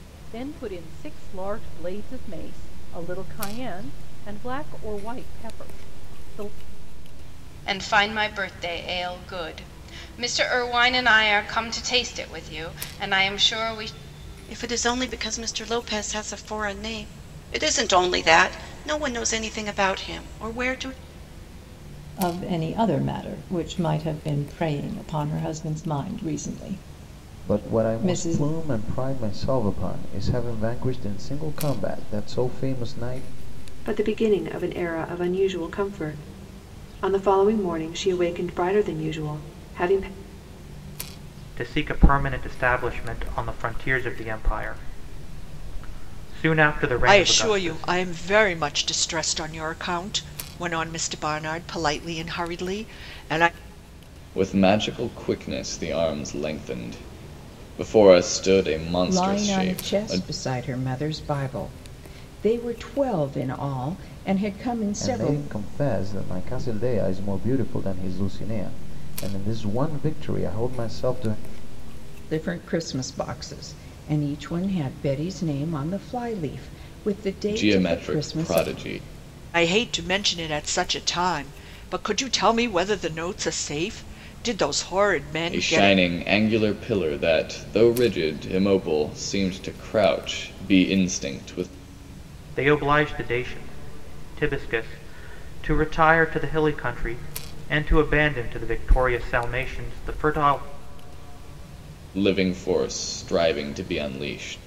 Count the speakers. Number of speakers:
10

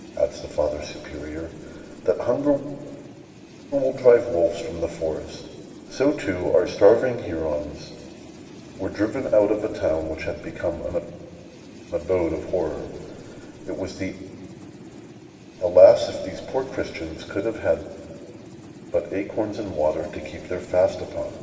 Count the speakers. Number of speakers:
1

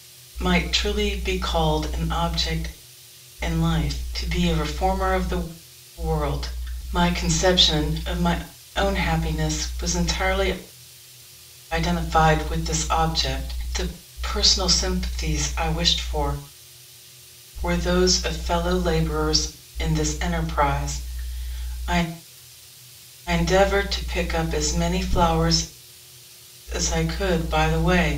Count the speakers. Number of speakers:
1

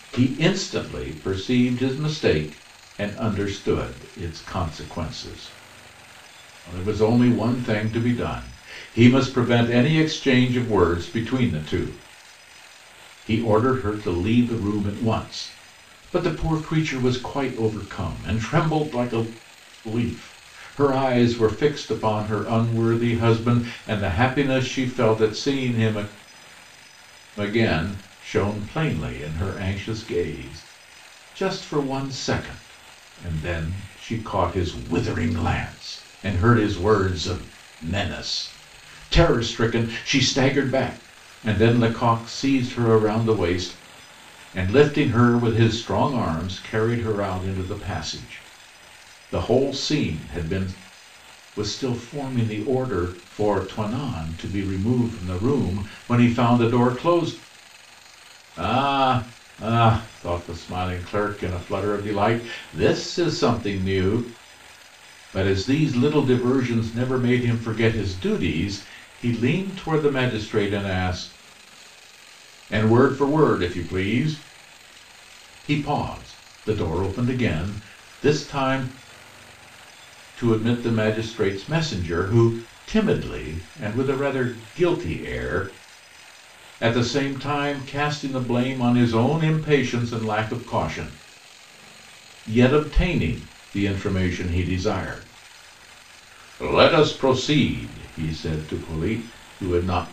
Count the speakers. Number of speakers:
1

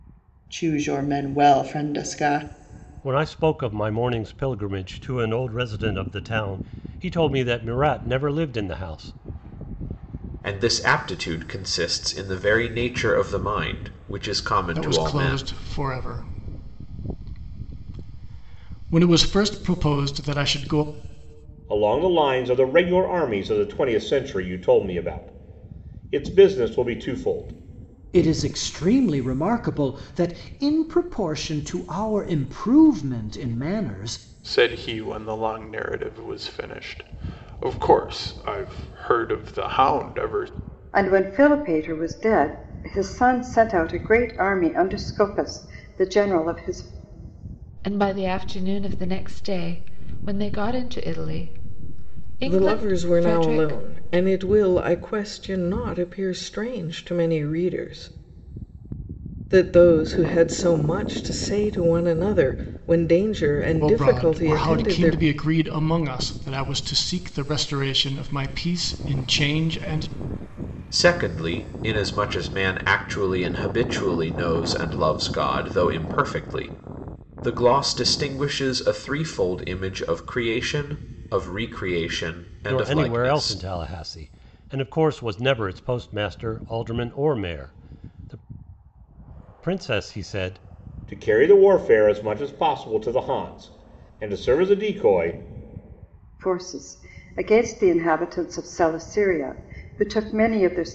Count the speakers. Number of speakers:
10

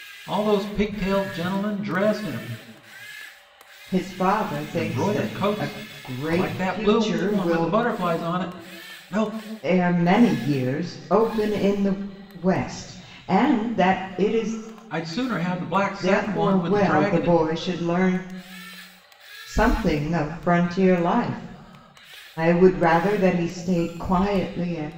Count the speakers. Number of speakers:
2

